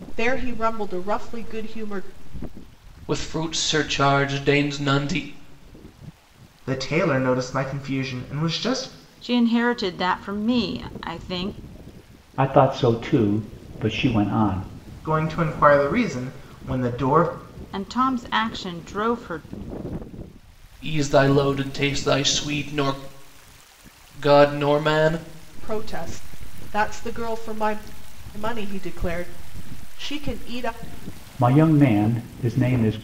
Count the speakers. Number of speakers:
5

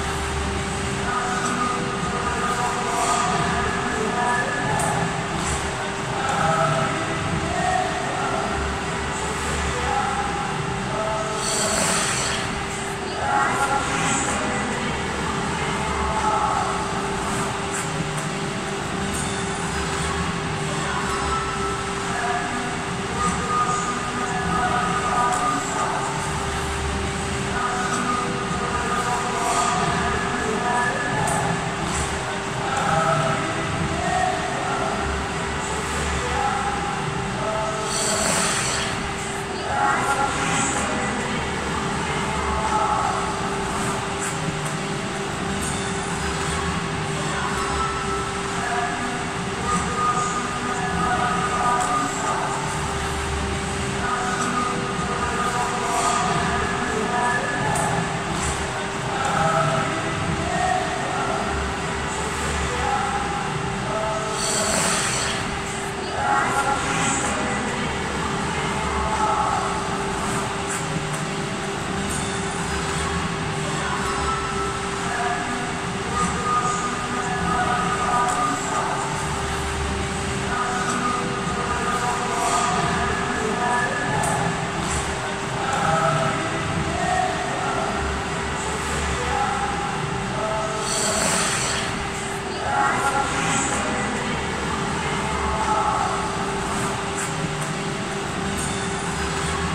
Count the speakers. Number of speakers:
0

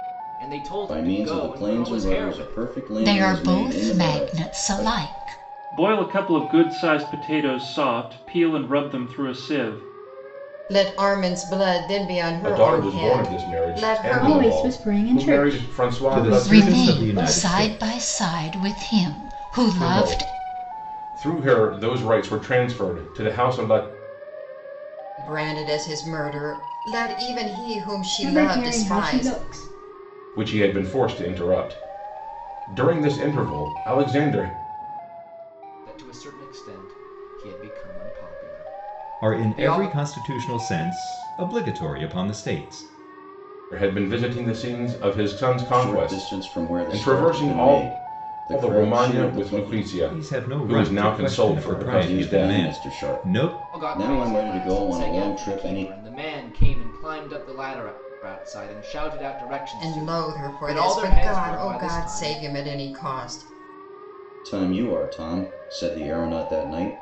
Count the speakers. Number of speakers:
8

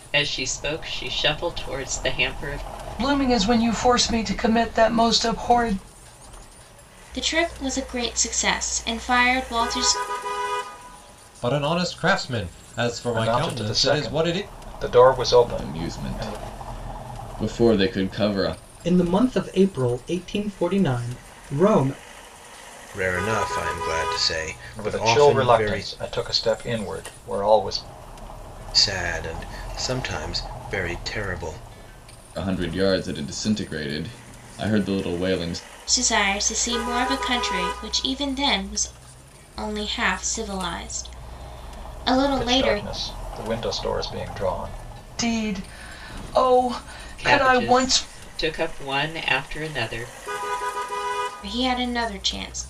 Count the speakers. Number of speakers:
8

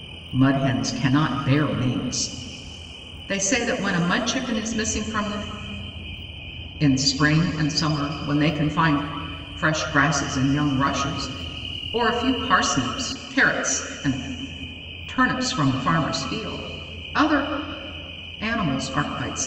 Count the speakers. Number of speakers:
1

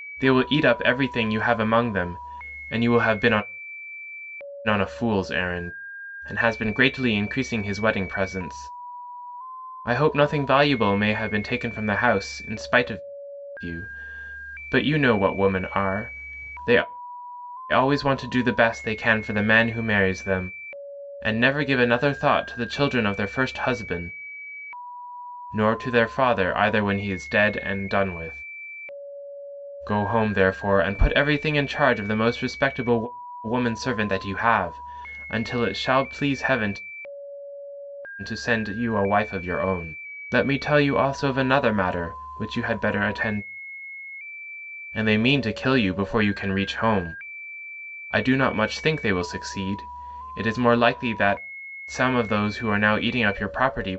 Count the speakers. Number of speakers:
1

